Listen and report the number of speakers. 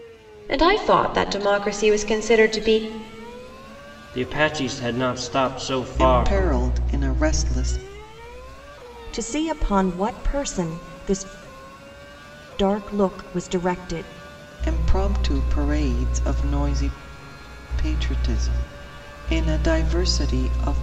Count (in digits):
4